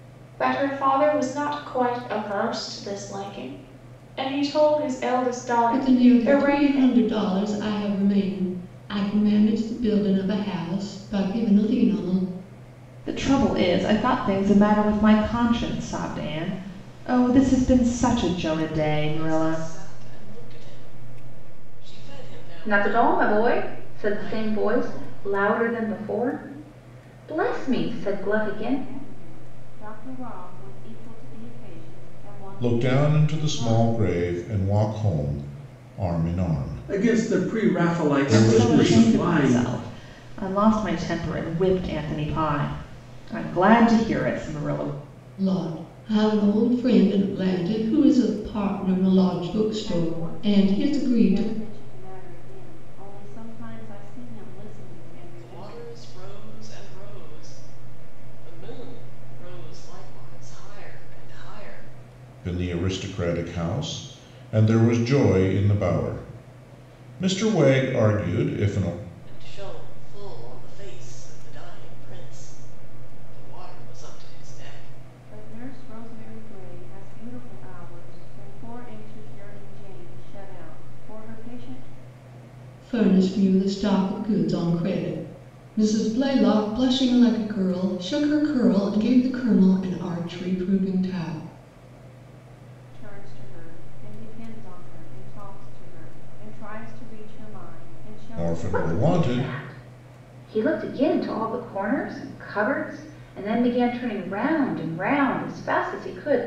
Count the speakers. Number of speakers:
8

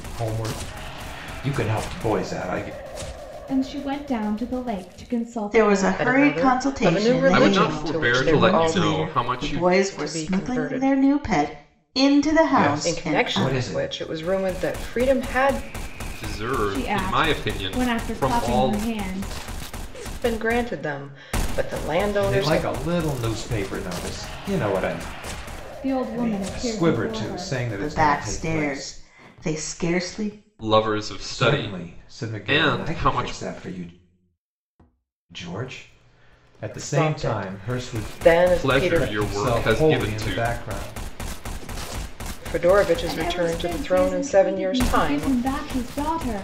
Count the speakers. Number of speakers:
5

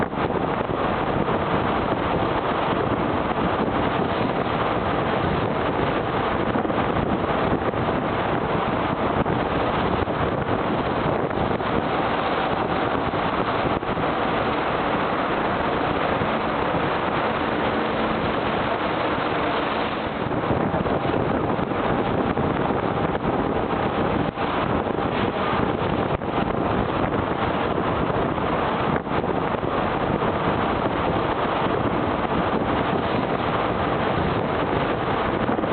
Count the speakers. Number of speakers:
0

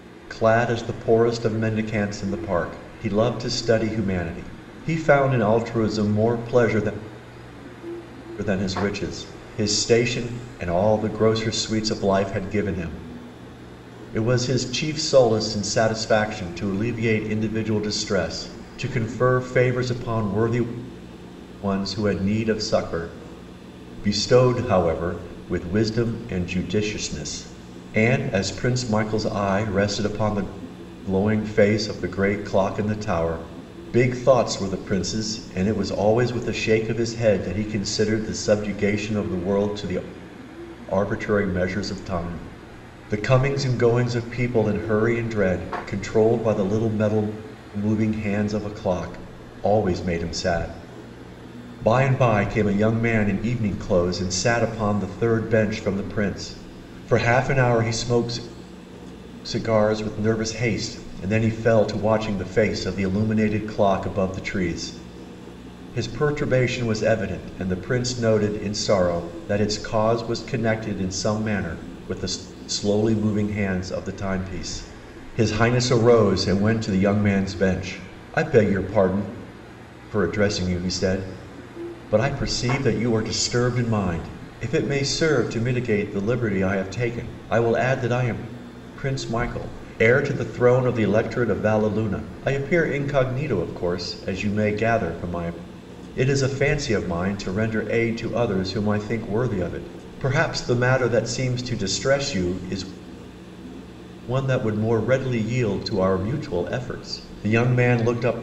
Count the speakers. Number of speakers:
1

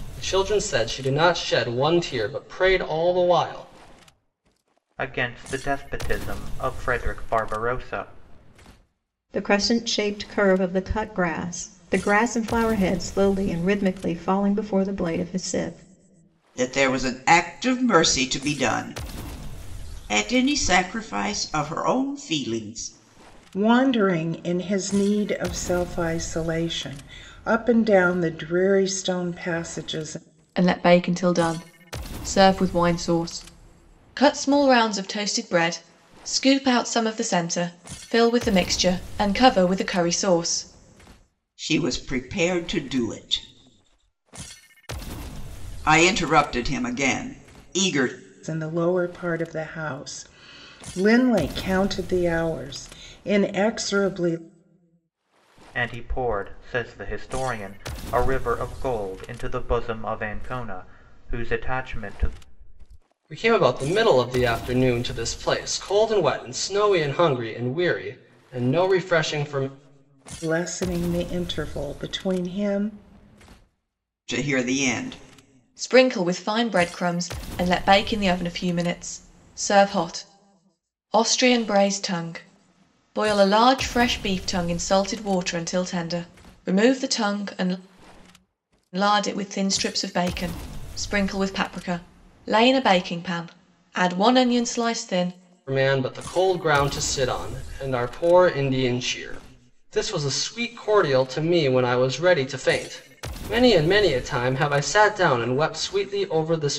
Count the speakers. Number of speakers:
6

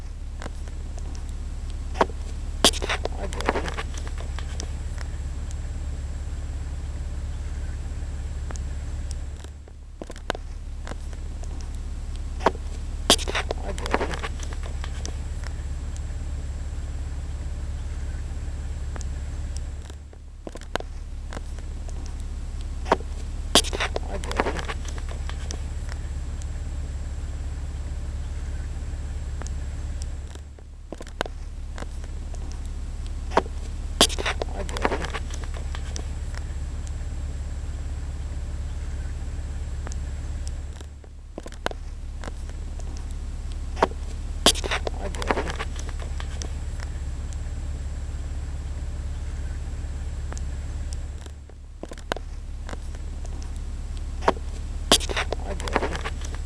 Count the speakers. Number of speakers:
0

